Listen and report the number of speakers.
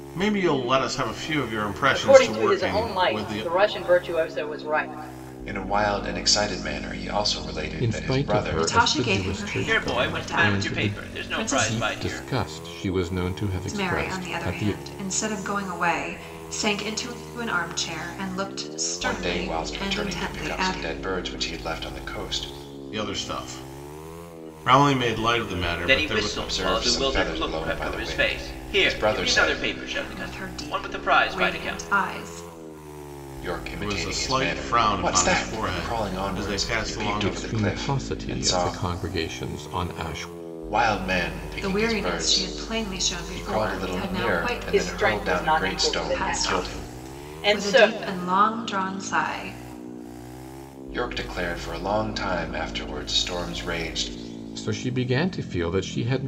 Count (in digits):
6